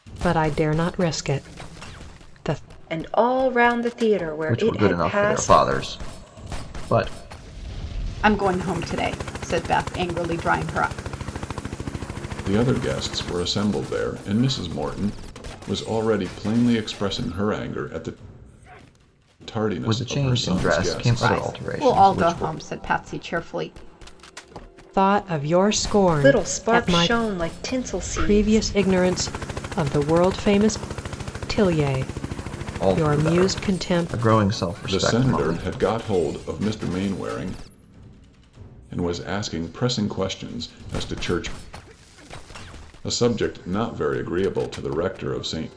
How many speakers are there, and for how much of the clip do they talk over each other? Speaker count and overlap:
5, about 17%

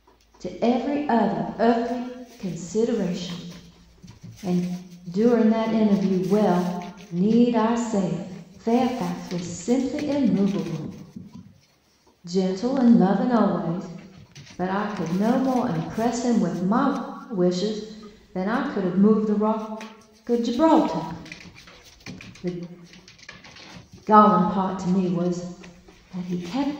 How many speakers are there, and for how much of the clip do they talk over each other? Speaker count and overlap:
1, no overlap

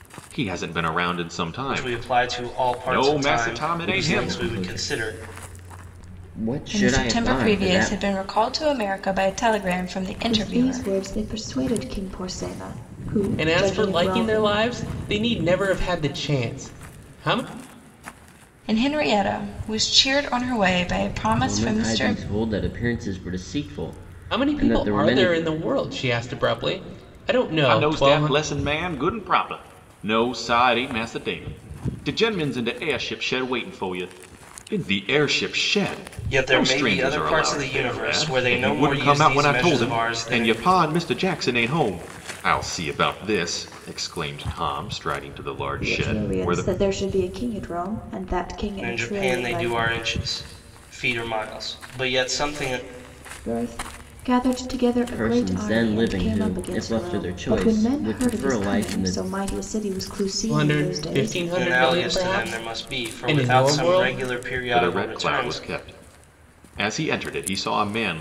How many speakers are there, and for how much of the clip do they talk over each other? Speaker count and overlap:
6, about 35%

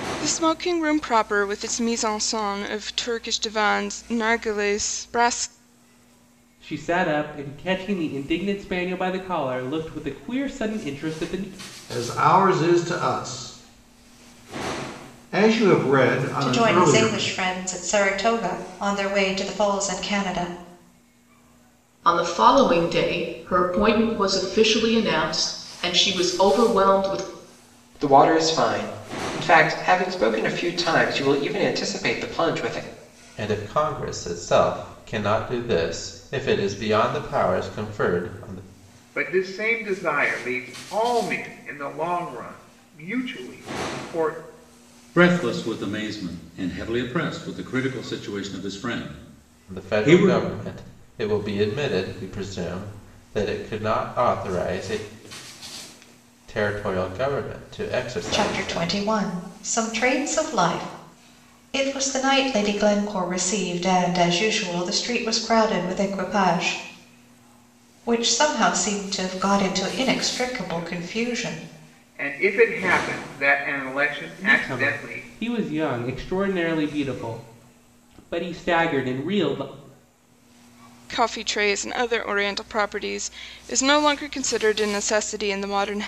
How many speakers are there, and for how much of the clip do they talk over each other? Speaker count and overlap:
9, about 5%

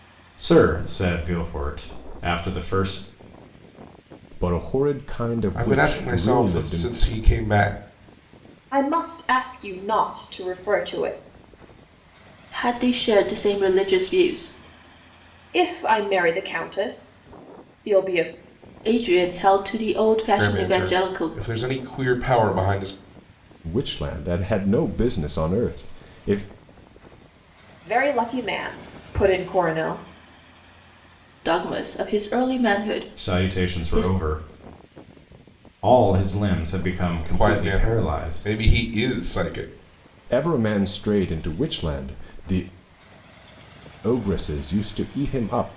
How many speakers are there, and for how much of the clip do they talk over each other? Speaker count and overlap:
5, about 10%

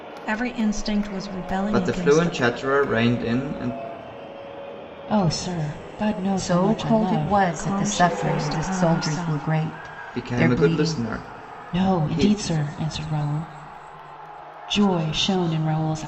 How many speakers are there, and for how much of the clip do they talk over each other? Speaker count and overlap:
4, about 34%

